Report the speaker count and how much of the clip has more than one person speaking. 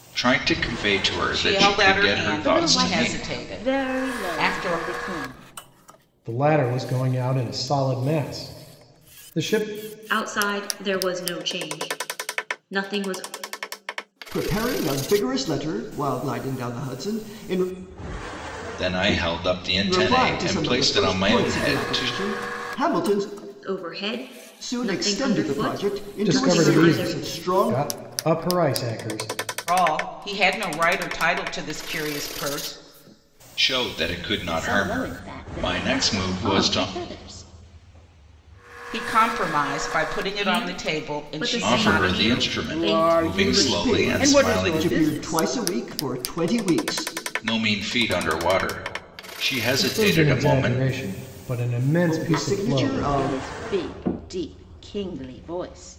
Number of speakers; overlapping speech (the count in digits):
6, about 34%